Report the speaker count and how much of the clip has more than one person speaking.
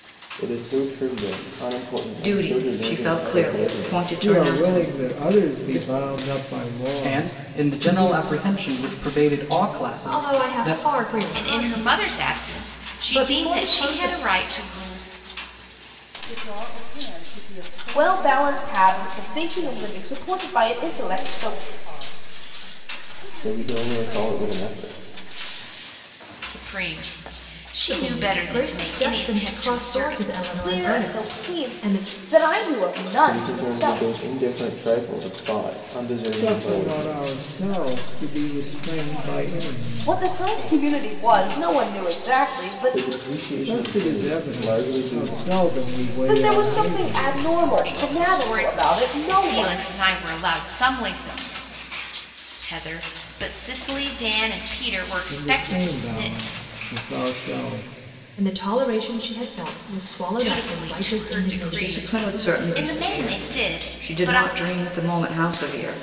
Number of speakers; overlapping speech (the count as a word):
eight, about 54%